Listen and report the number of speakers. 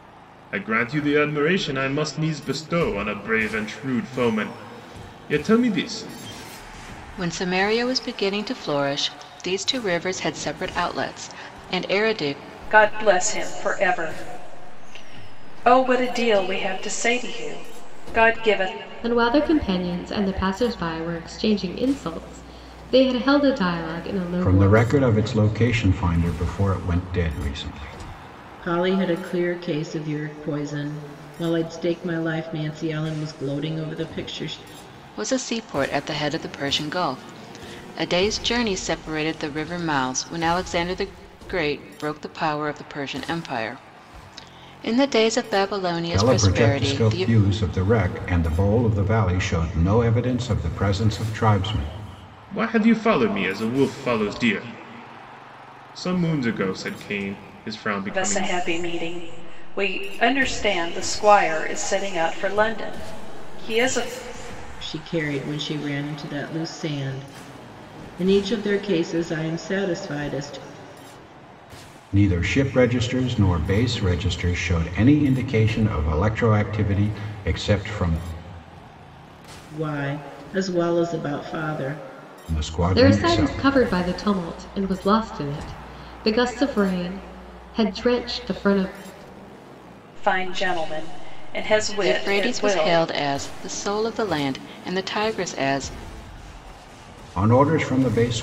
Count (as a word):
six